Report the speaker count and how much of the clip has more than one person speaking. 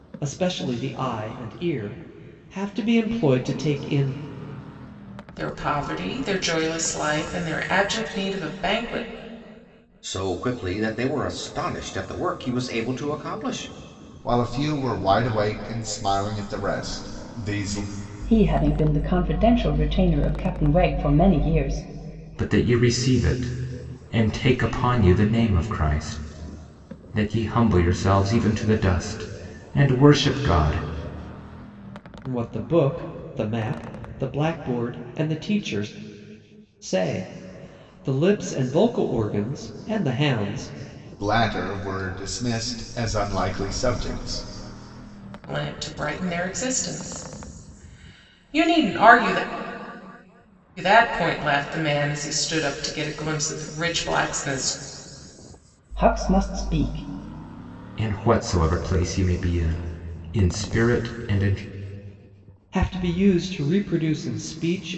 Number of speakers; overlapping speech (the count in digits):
6, no overlap